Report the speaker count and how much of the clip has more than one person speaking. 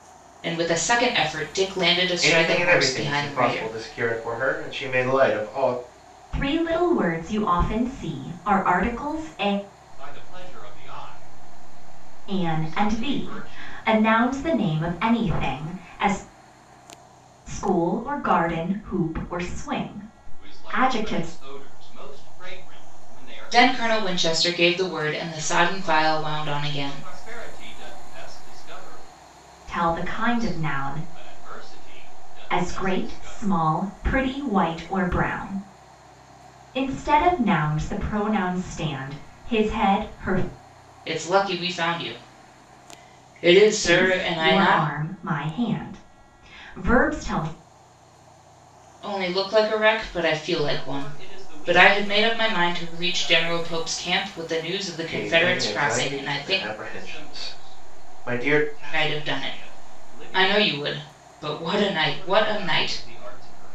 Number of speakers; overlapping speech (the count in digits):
4, about 31%